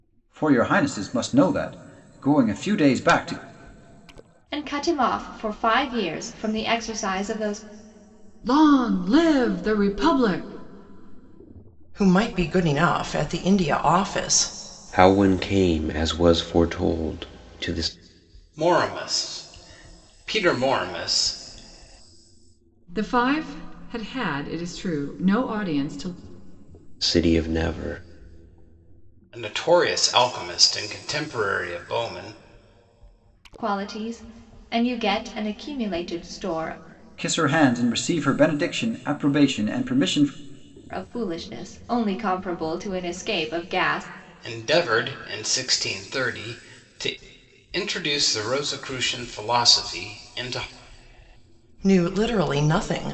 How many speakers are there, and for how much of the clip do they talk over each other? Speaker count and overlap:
6, no overlap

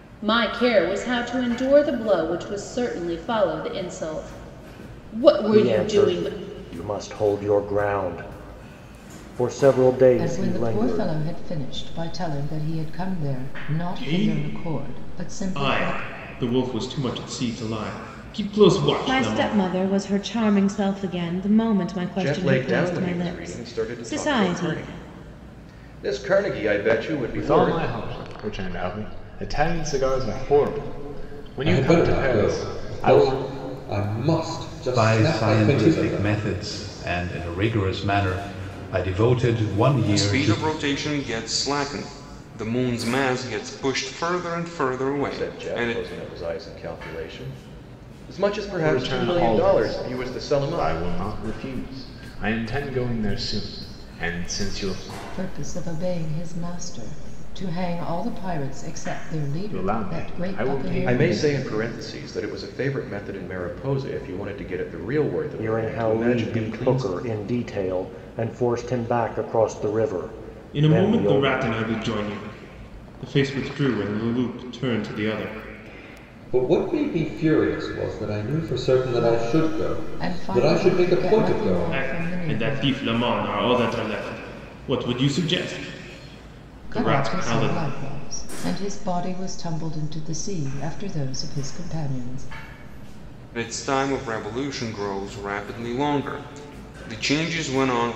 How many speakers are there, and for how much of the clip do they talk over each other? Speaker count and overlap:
10, about 24%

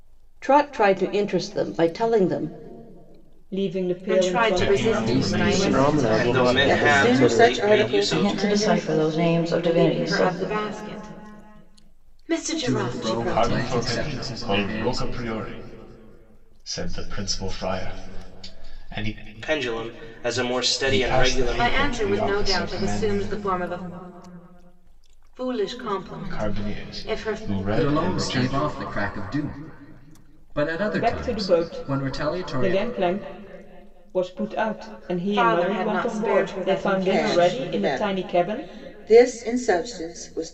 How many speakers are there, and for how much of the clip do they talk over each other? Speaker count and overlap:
9, about 45%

